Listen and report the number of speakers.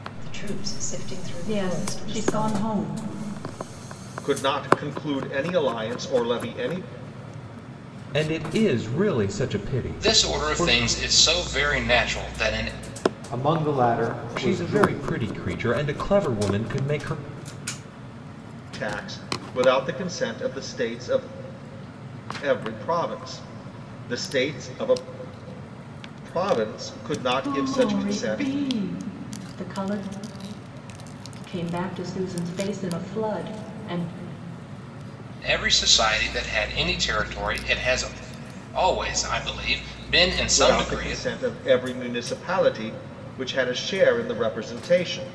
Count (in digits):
6